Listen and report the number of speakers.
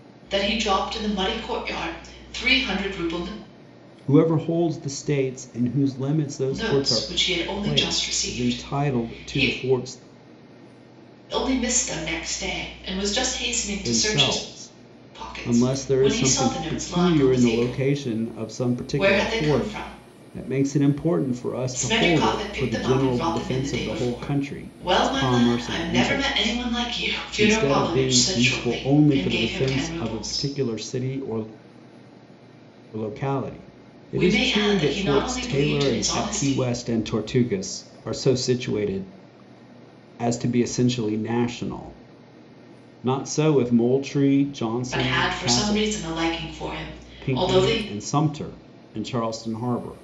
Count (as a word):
two